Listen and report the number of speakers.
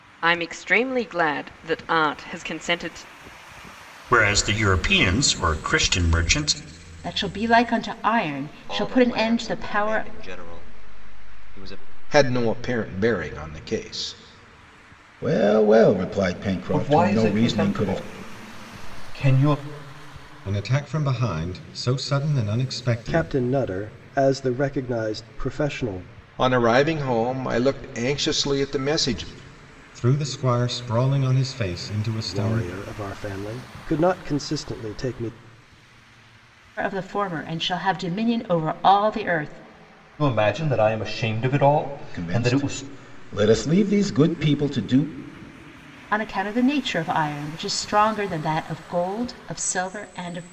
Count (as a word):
nine